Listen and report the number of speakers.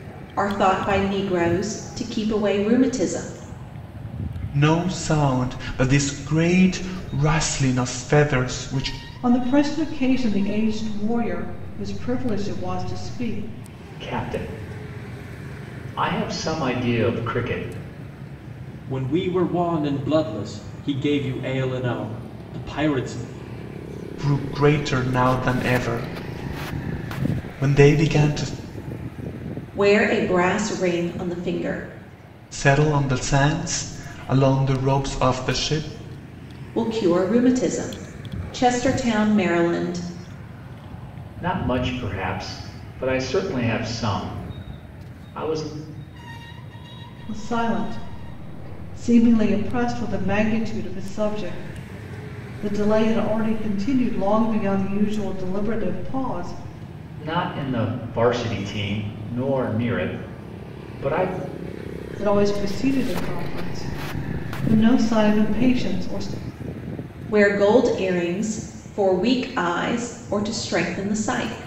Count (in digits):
5